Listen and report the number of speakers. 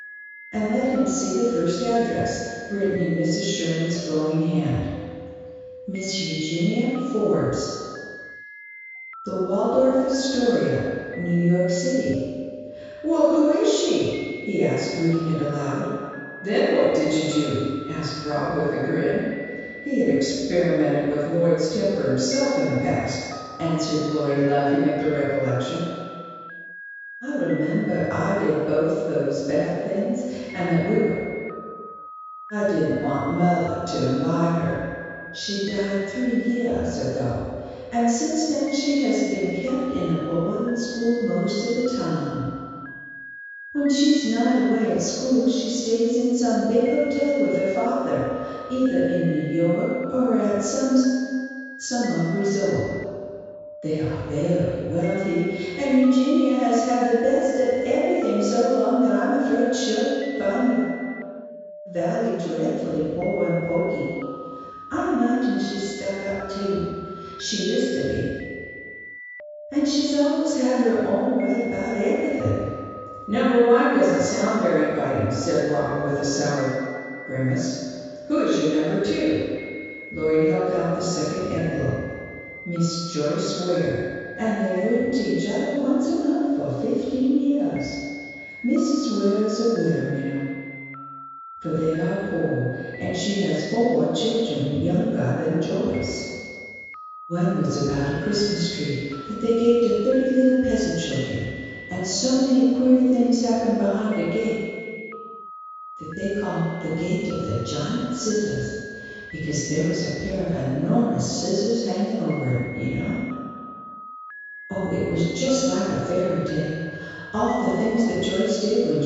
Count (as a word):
one